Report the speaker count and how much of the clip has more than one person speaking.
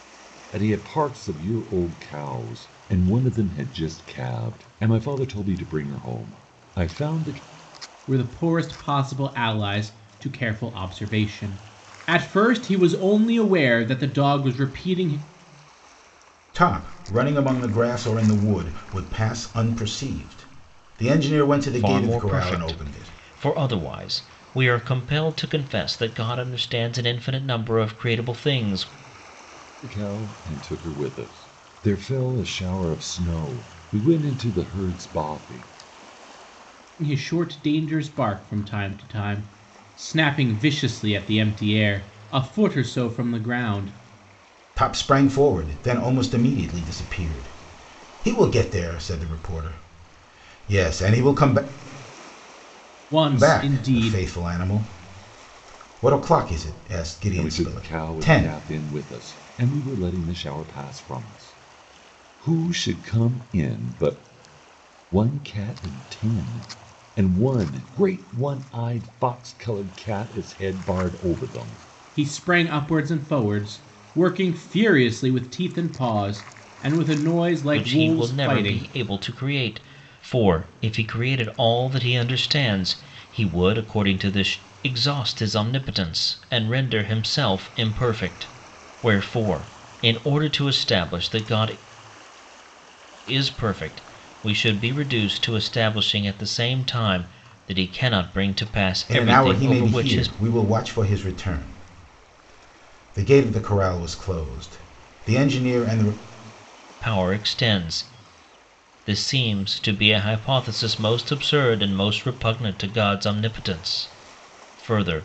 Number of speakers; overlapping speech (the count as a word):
four, about 5%